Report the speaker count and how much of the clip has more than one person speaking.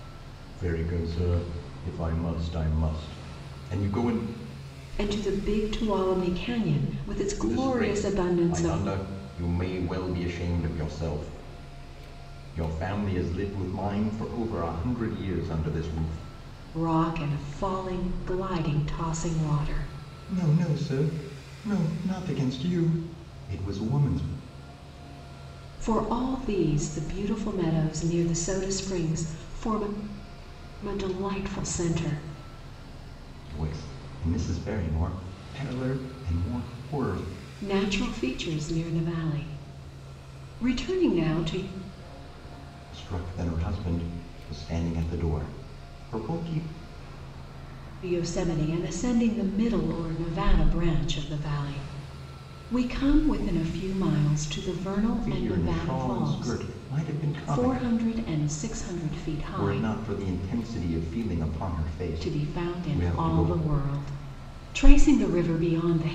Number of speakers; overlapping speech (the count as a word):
two, about 8%